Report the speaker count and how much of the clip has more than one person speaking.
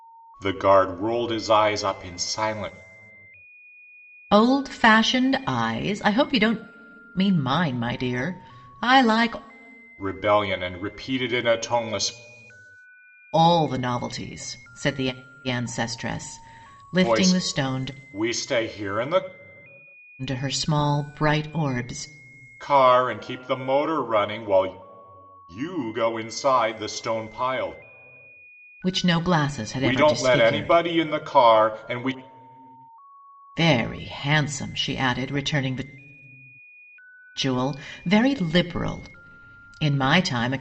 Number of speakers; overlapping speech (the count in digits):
2, about 5%